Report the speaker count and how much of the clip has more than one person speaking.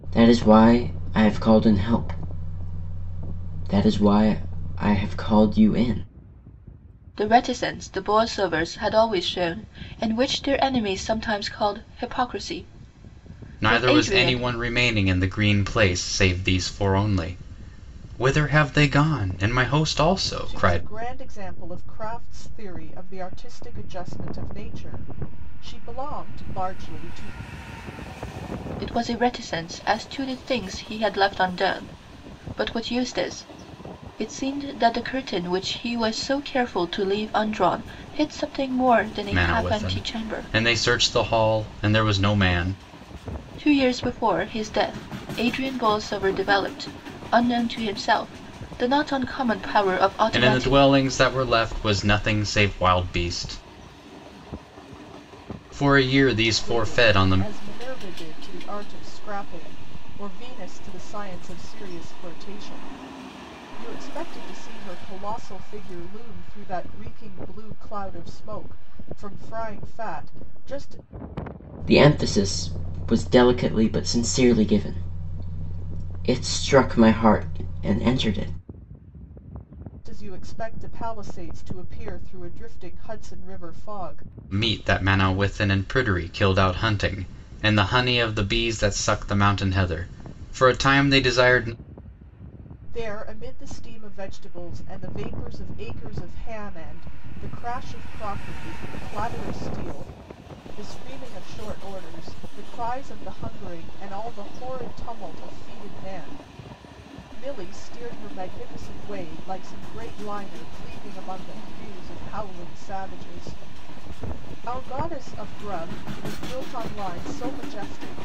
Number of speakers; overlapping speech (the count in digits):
4, about 3%